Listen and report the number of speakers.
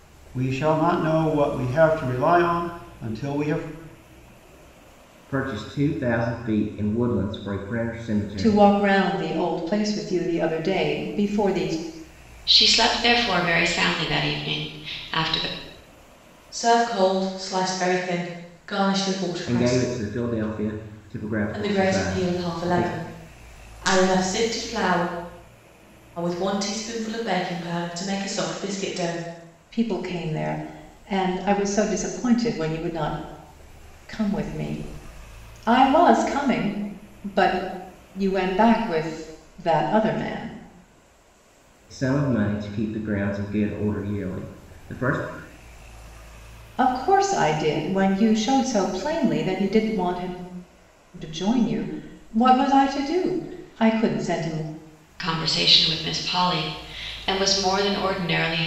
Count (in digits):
5